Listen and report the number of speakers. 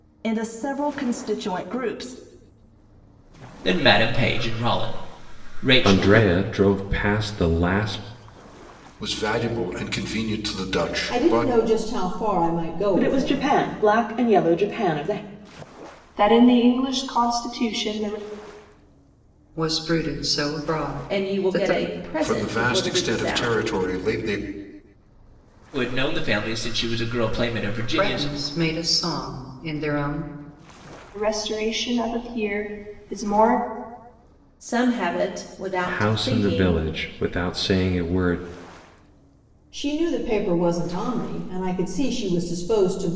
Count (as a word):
nine